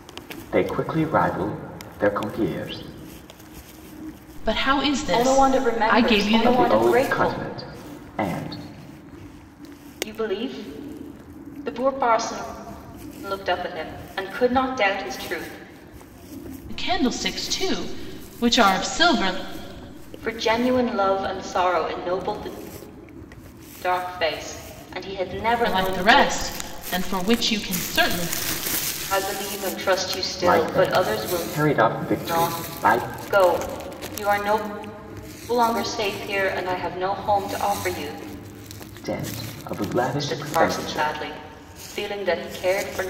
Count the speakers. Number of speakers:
3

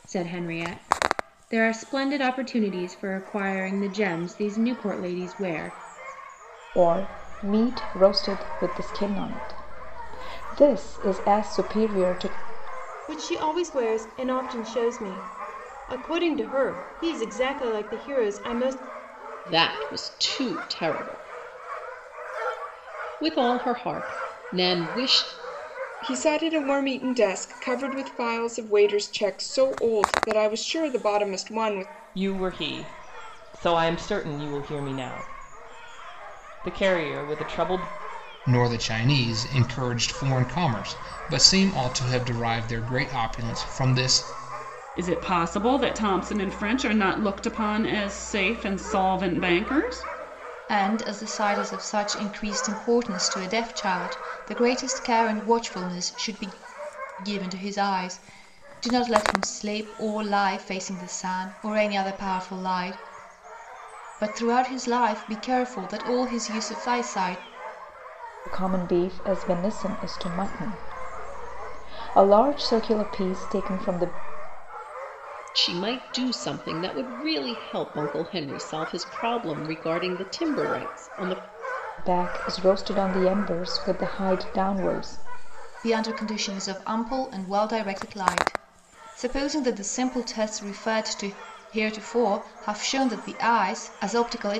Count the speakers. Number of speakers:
9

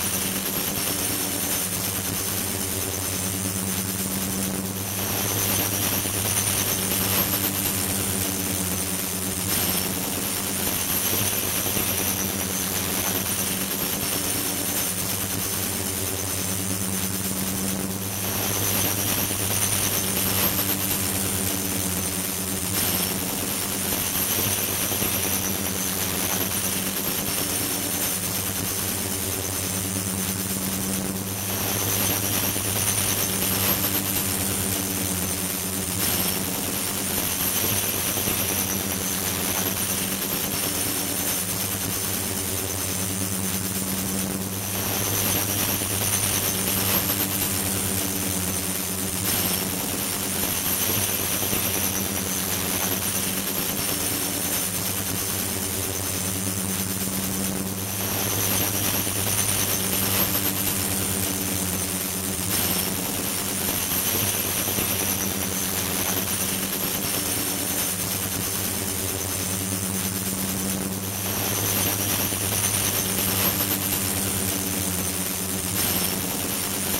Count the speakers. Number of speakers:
0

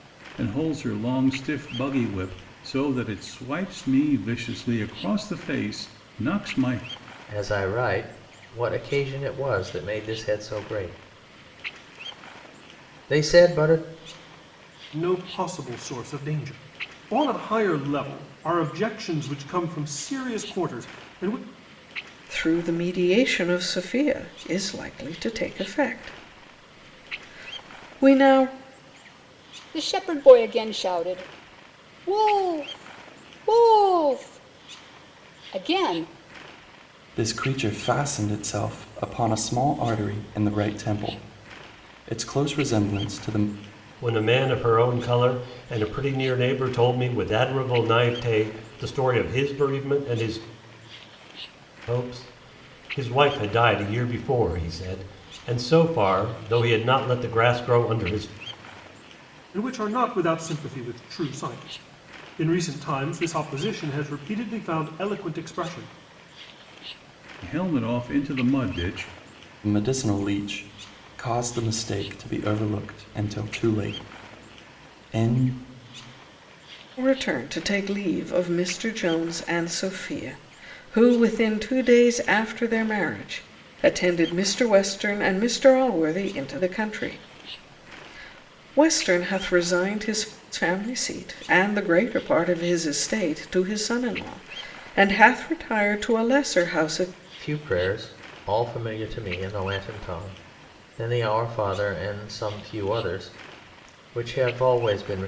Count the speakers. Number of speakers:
7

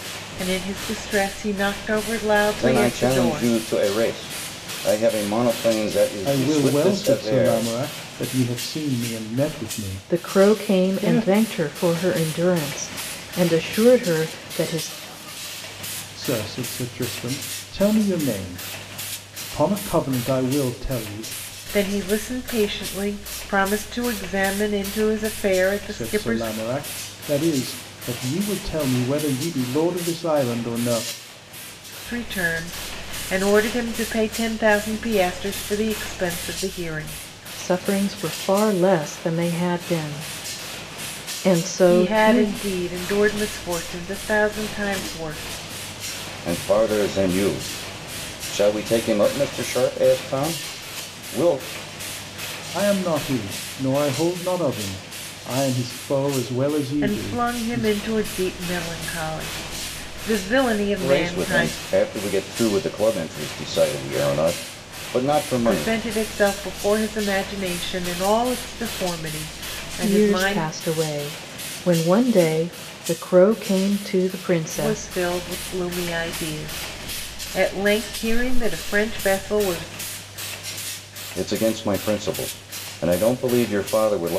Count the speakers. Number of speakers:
4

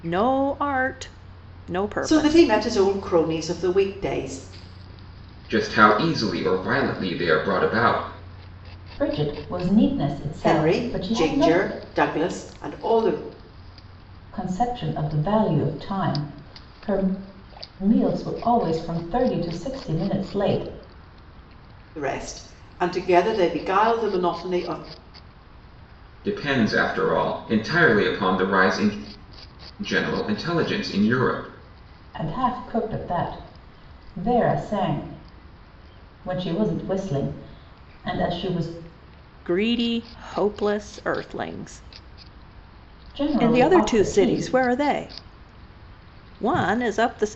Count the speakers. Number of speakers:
4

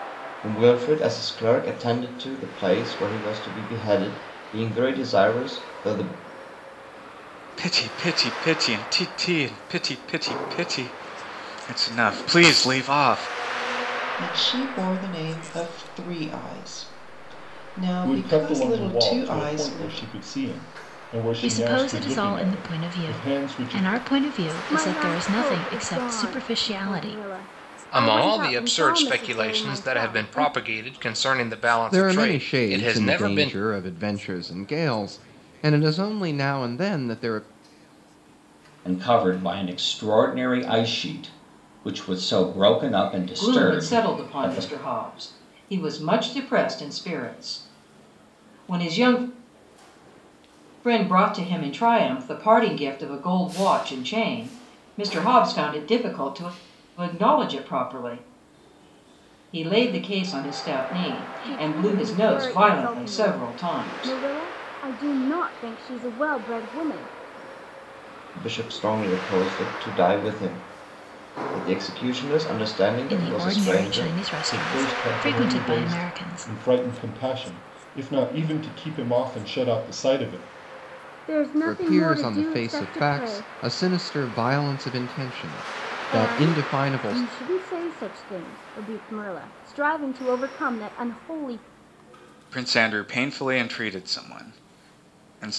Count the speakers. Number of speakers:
10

